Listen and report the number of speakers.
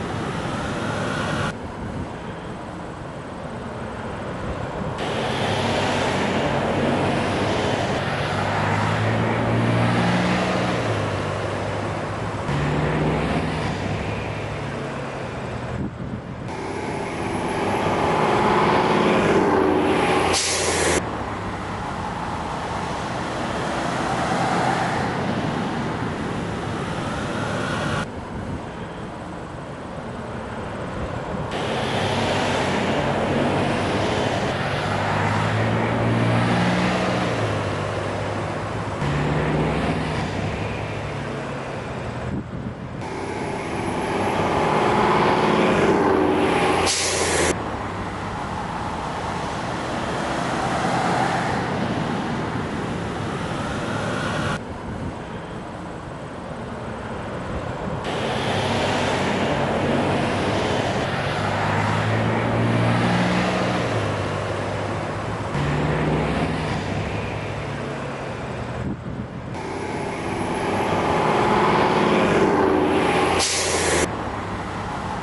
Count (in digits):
0